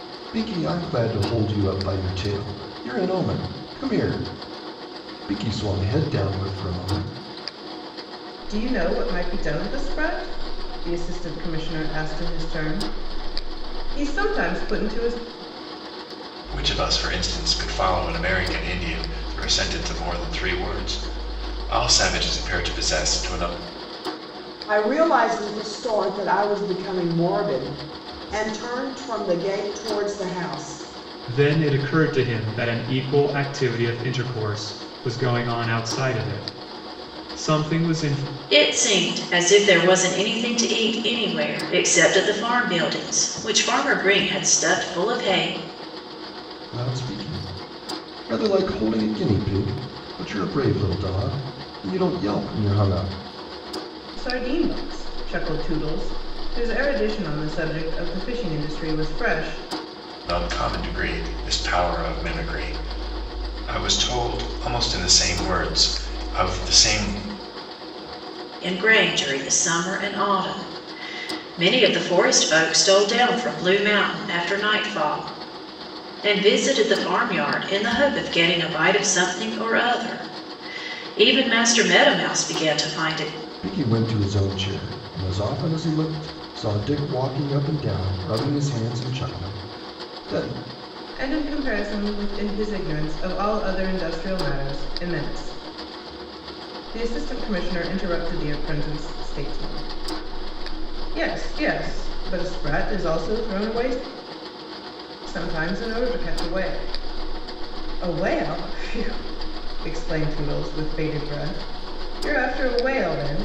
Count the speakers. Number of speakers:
6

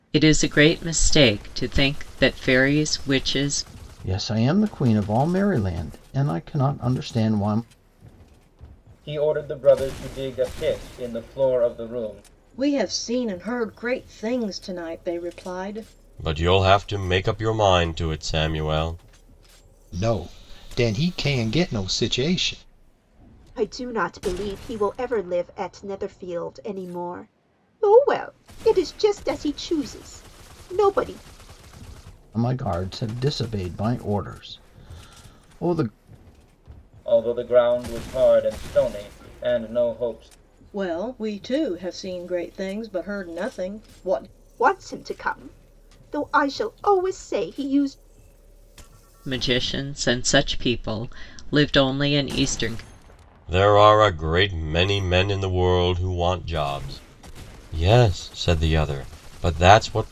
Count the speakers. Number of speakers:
7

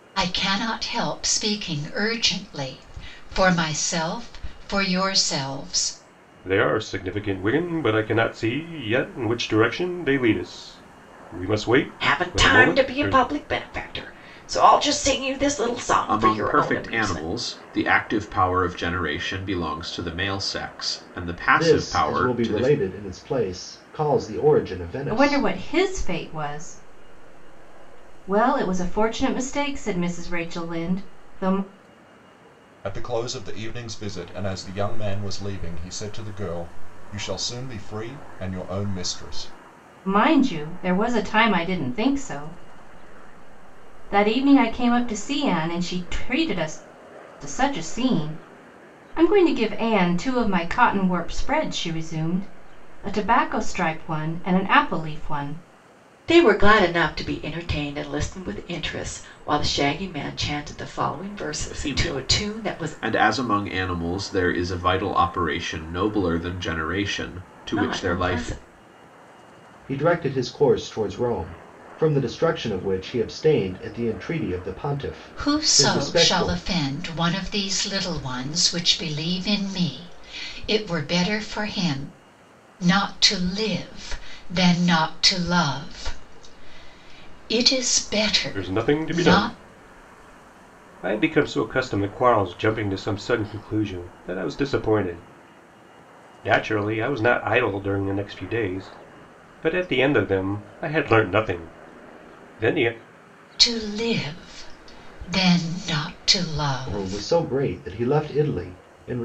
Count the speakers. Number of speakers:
7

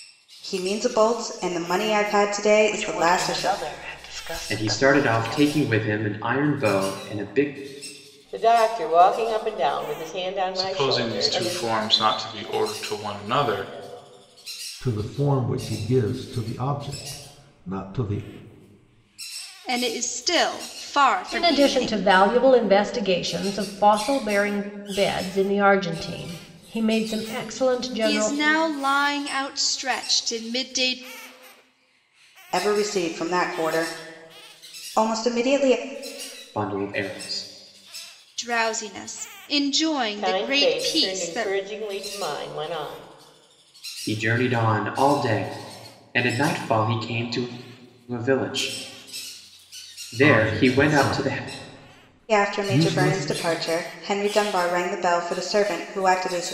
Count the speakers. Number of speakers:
8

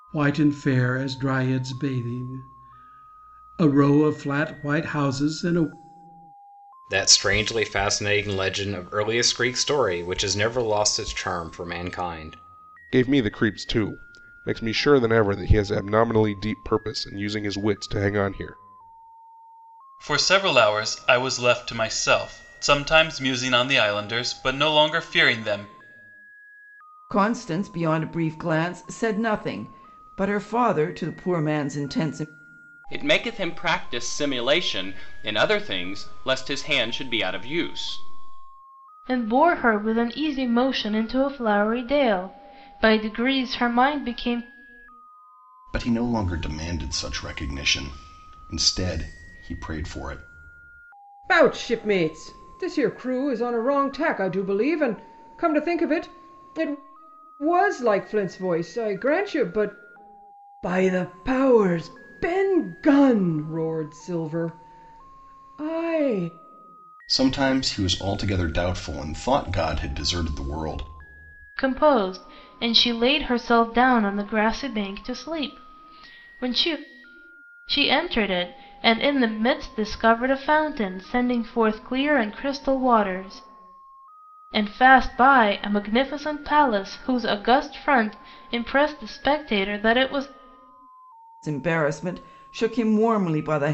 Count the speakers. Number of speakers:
9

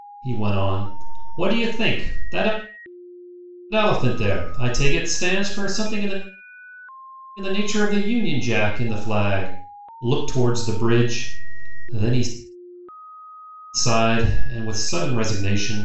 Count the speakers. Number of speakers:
1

